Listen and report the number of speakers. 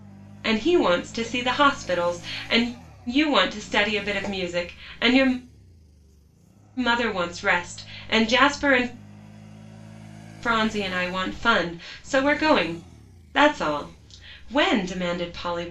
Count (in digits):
1